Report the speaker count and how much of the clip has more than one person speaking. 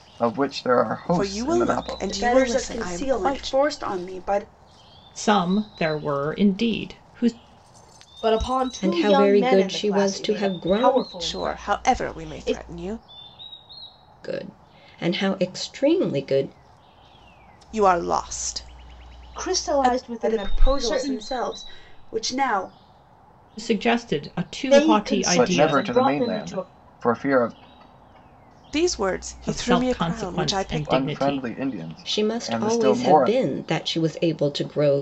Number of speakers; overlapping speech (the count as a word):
six, about 38%